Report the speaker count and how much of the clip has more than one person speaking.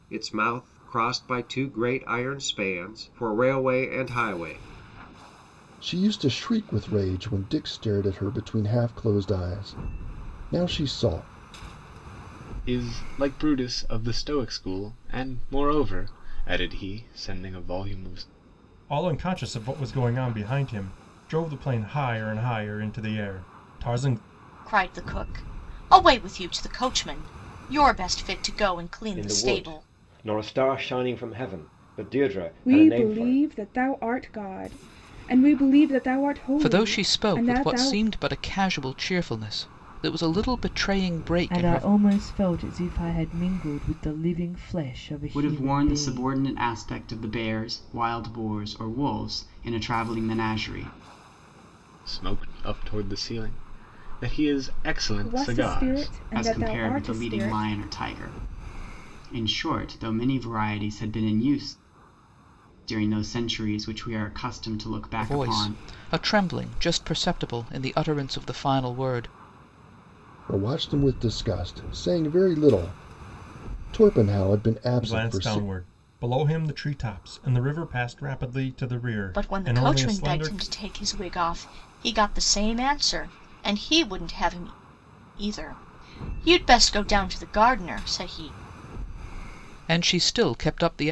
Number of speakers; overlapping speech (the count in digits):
10, about 11%